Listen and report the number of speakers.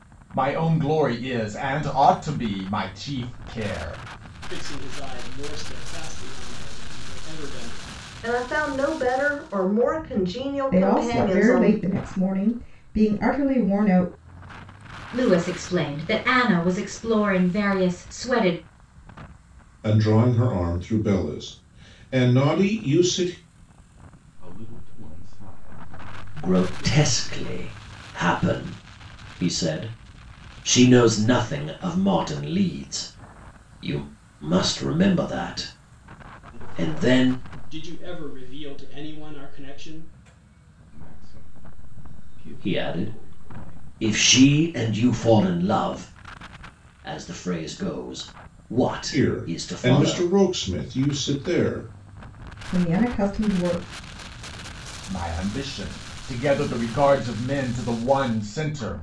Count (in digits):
8